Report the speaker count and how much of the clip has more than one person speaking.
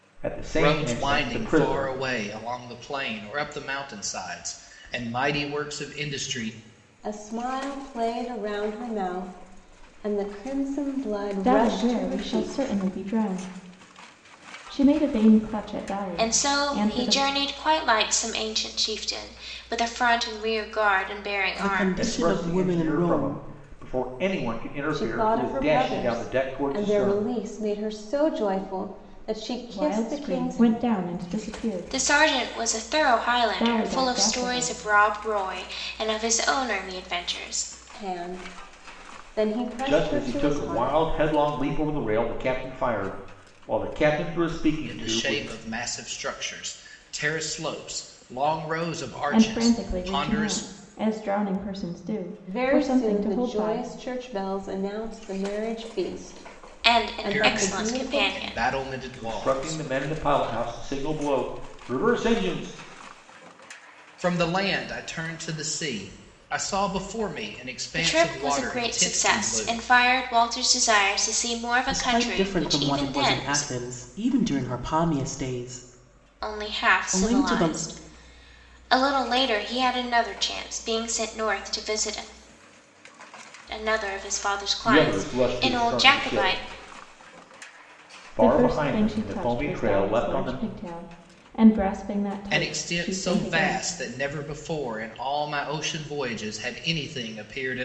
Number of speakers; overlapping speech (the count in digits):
6, about 31%